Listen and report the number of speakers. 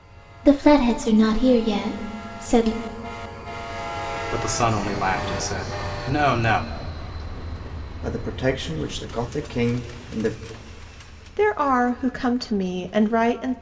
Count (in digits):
4